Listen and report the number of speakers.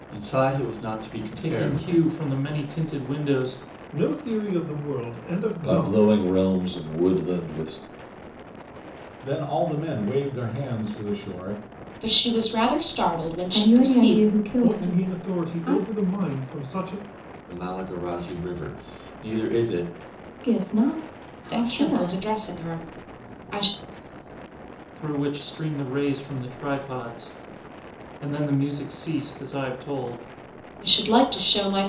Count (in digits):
7